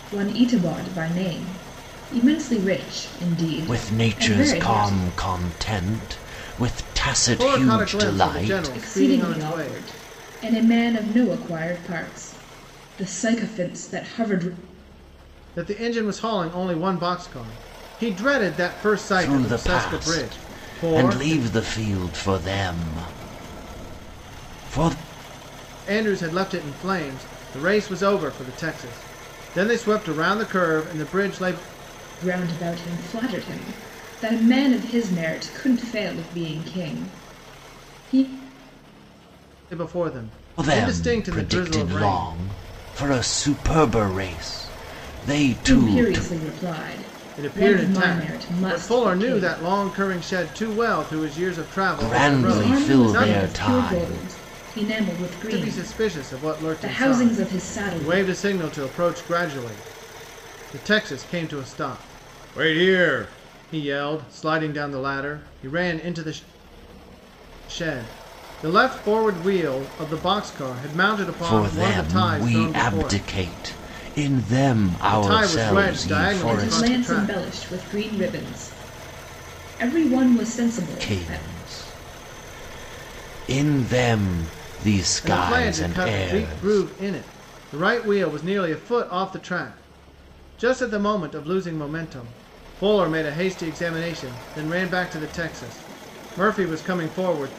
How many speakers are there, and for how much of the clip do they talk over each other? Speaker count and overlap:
3, about 23%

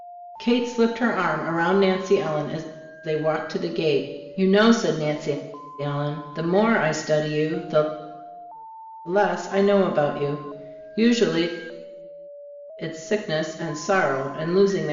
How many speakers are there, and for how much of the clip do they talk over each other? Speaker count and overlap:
1, no overlap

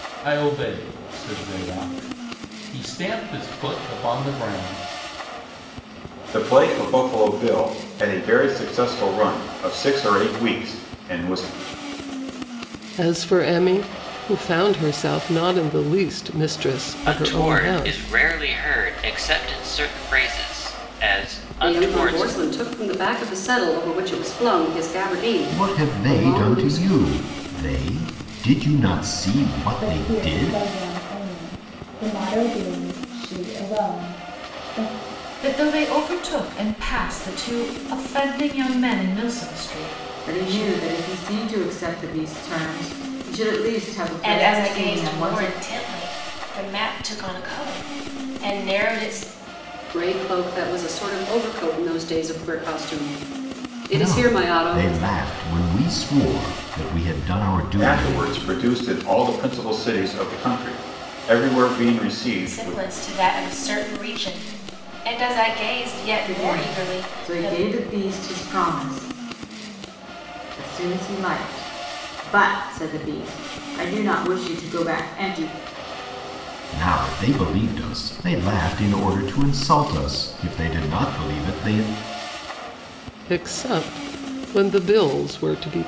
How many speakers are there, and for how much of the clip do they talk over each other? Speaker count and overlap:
10, about 11%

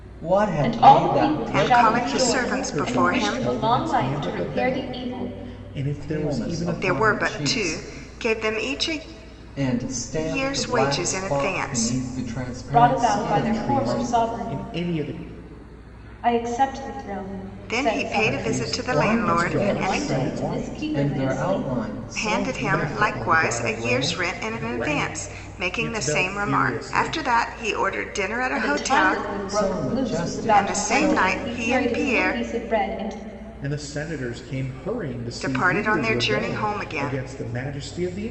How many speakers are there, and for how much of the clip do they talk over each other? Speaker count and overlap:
4, about 64%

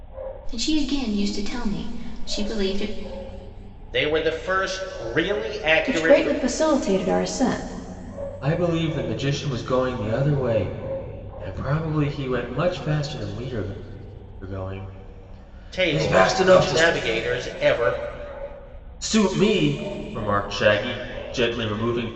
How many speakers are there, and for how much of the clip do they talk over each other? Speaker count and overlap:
4, about 8%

